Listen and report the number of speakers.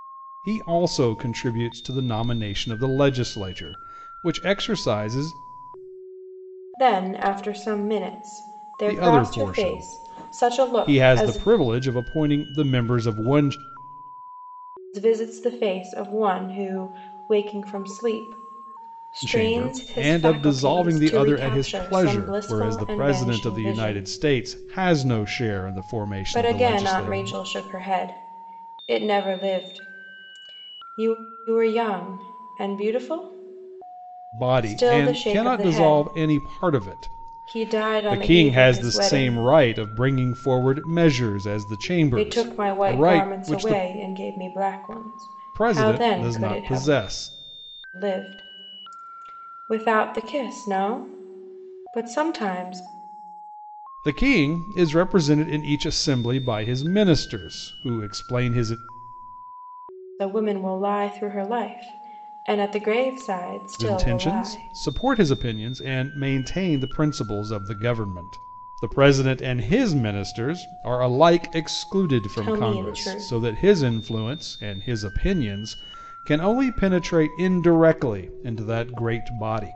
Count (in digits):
2